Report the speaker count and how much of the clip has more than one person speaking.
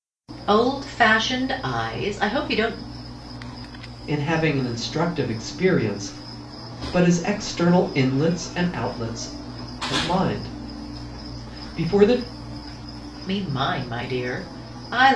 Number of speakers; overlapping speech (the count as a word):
two, no overlap